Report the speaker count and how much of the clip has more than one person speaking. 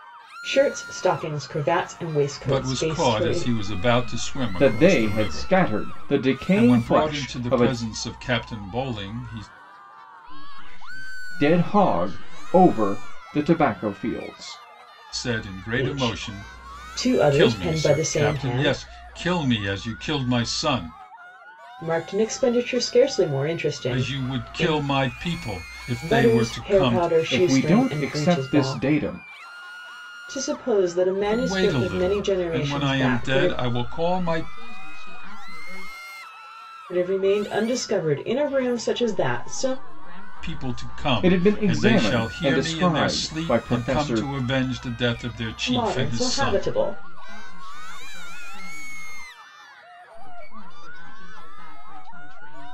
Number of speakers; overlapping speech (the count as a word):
four, about 43%